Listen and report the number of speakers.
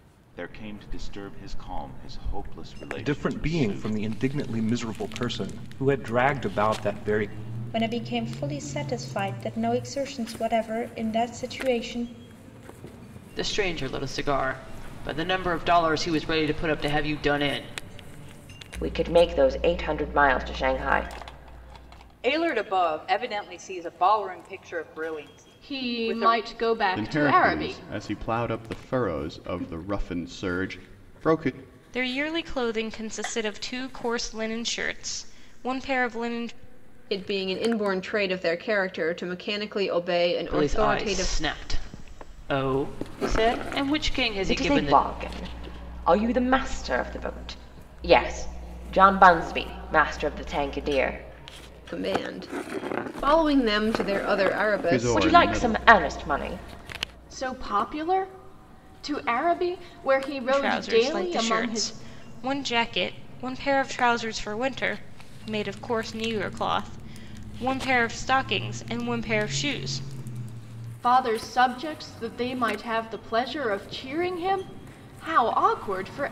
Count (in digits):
10